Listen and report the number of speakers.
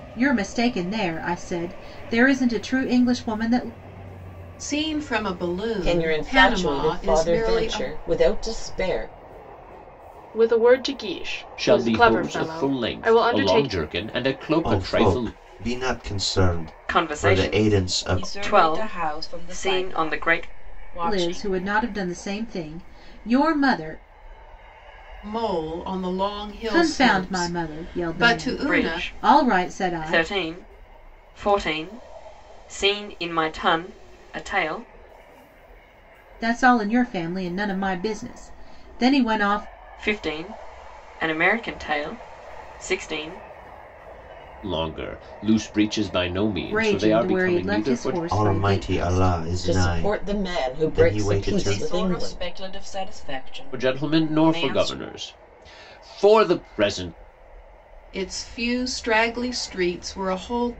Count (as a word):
eight